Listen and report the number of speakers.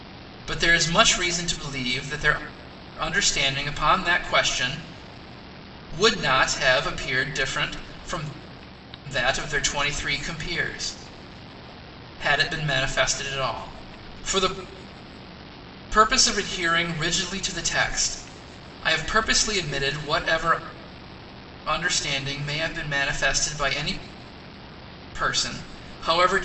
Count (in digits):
1